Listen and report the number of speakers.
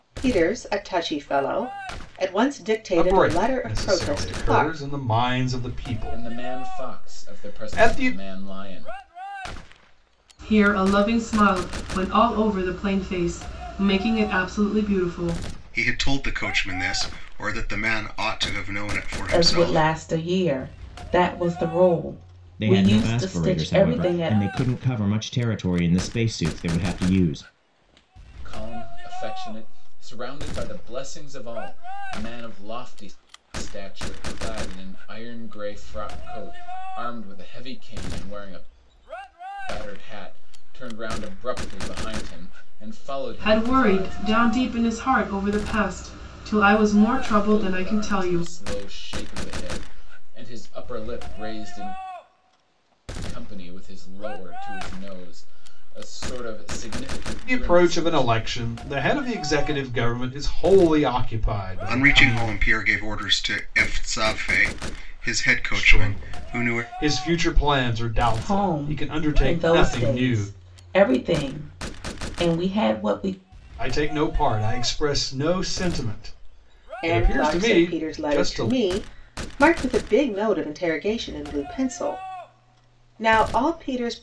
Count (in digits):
7